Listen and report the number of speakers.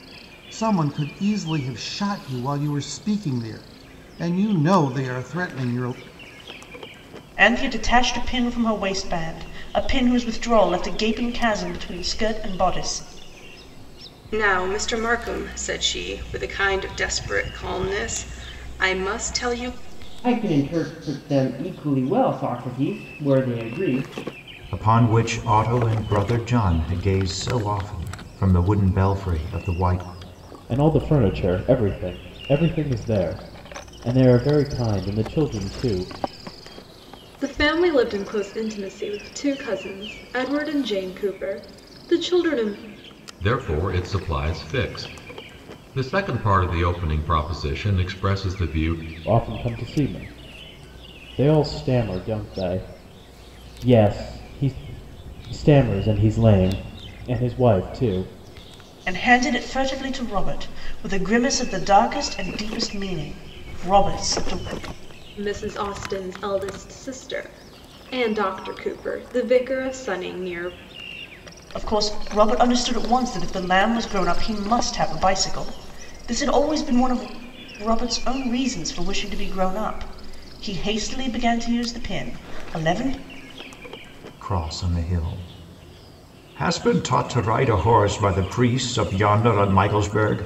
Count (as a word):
eight